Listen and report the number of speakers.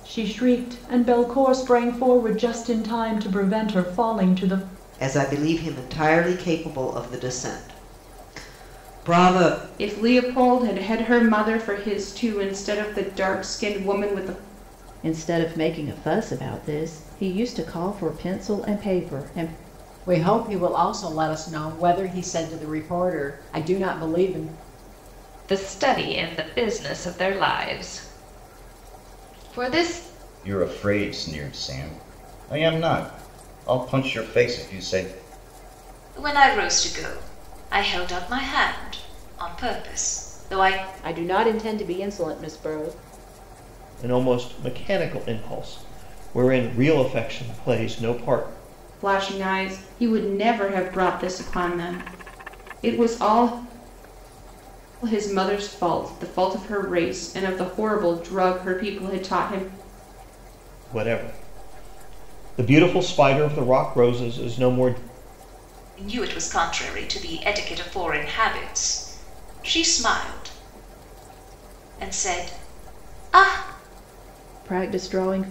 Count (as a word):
ten